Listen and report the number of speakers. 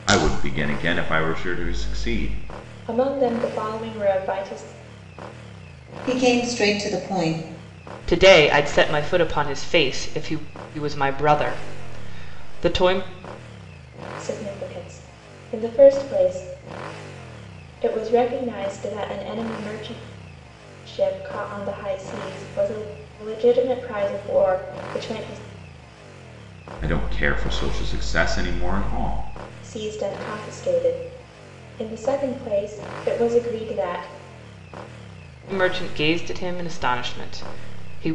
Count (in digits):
4